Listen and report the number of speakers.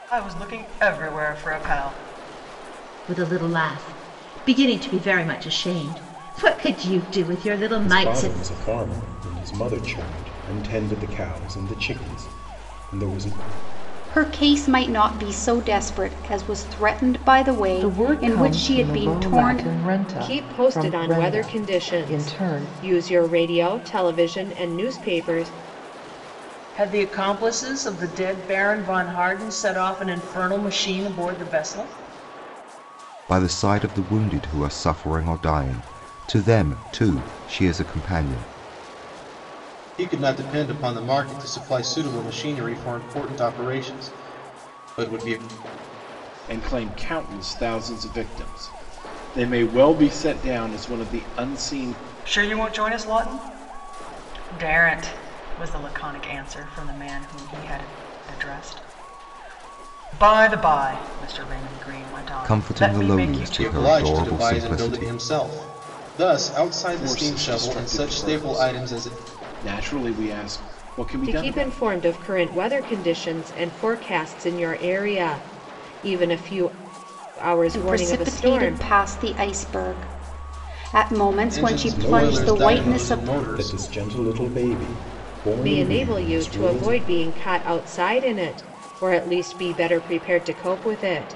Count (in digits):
10